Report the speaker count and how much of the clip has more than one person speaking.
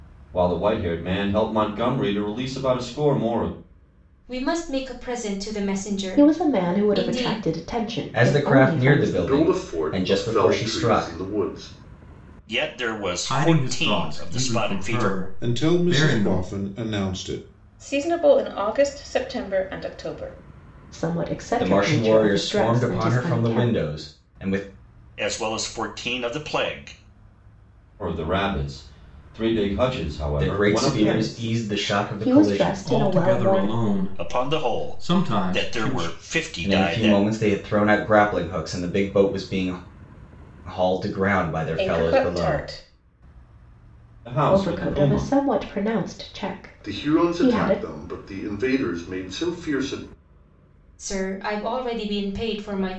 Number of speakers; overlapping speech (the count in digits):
9, about 35%